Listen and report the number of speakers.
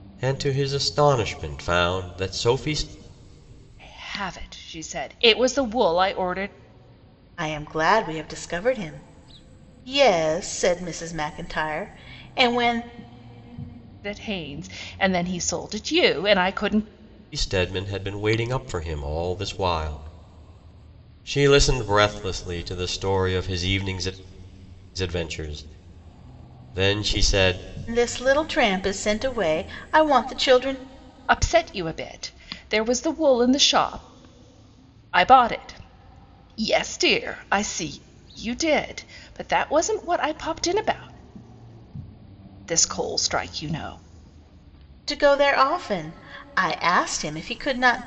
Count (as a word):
three